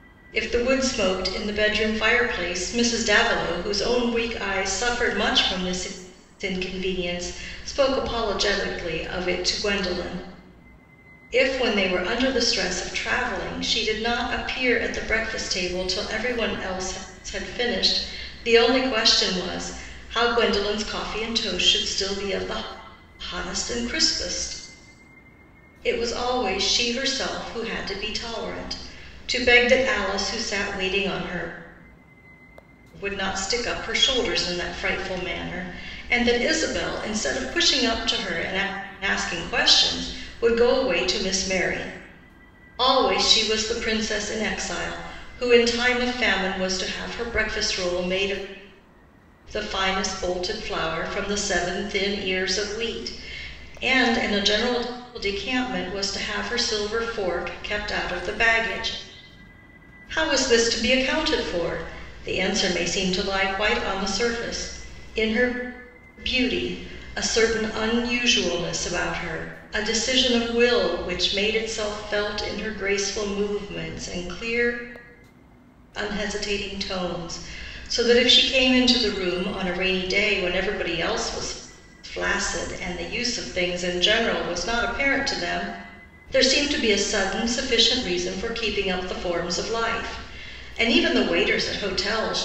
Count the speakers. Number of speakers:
1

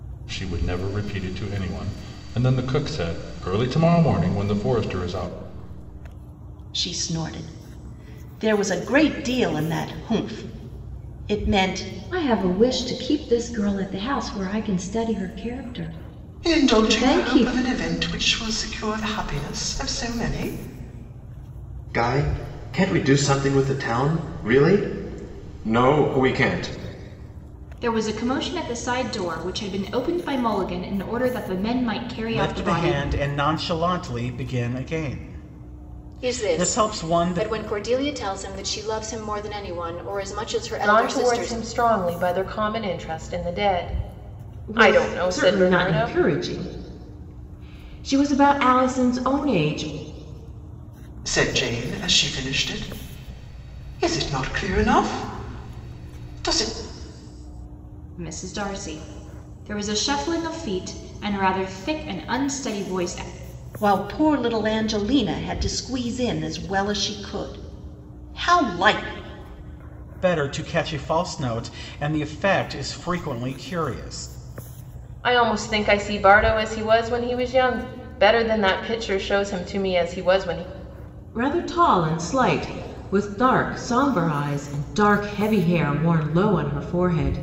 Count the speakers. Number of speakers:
10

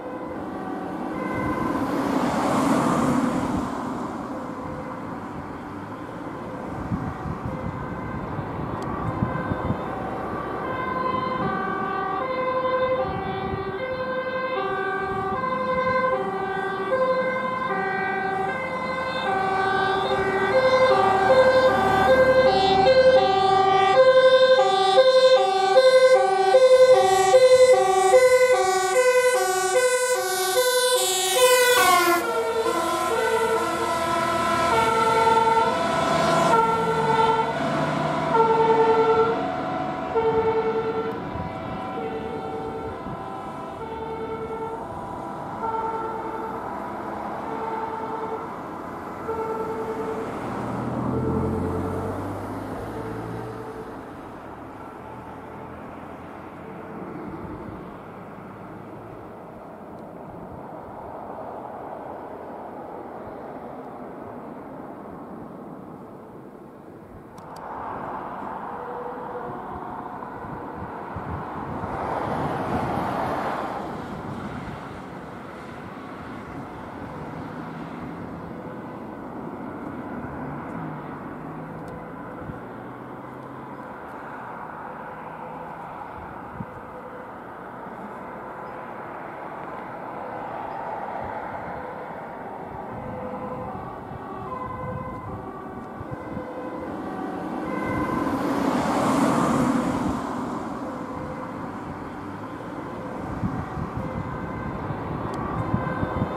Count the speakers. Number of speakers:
0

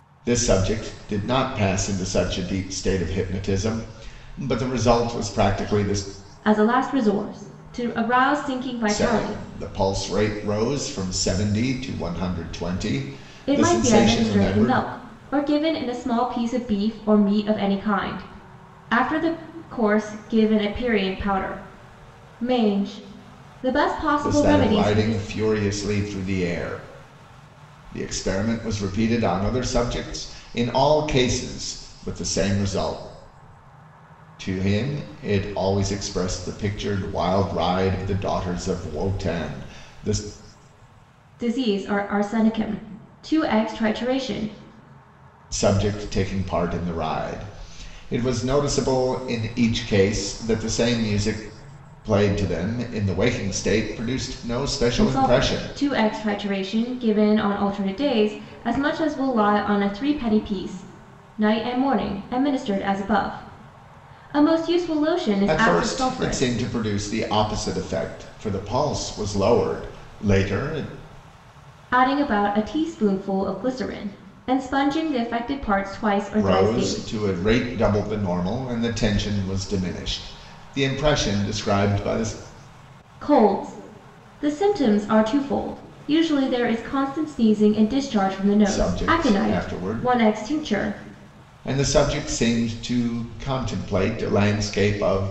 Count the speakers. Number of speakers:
2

